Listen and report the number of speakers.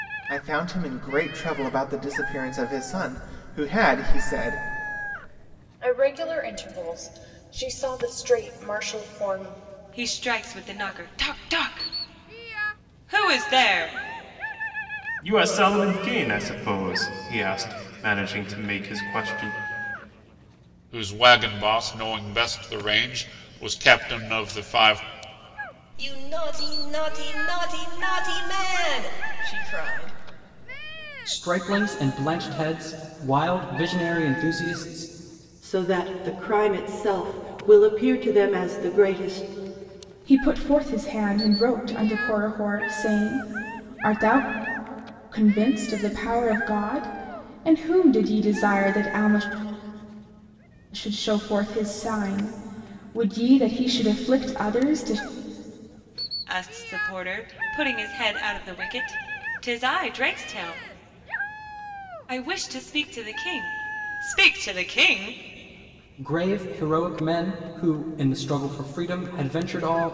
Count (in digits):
9